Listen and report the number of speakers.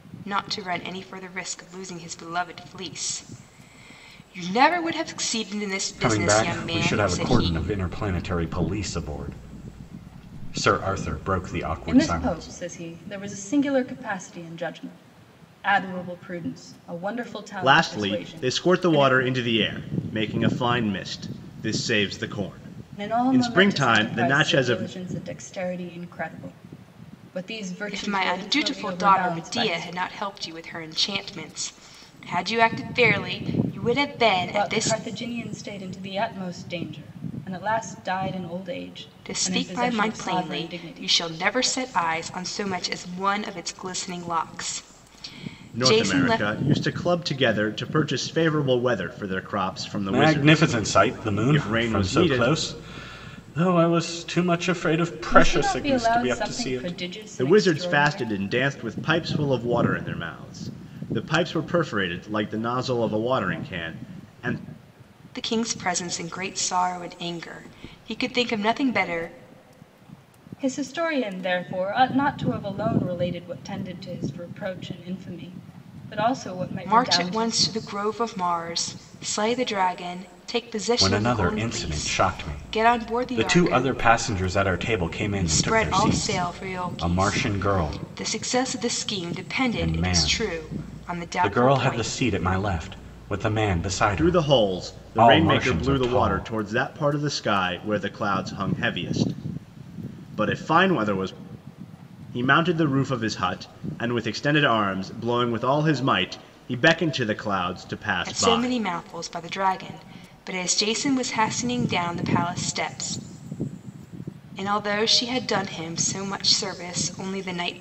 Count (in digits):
4